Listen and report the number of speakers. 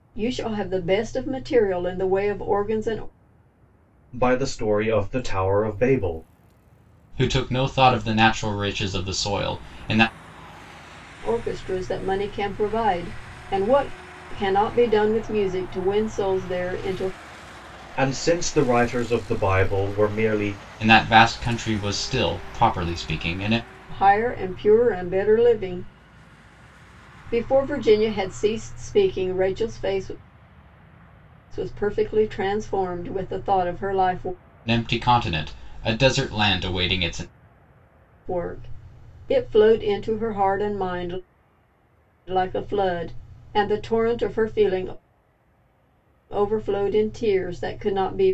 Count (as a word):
three